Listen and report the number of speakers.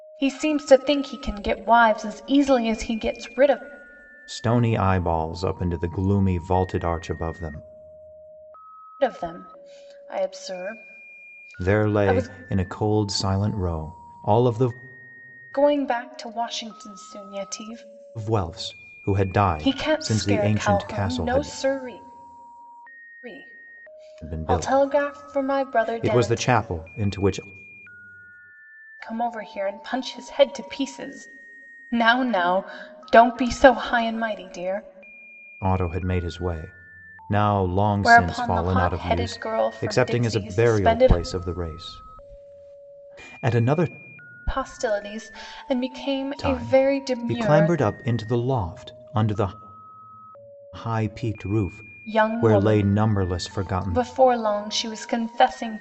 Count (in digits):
2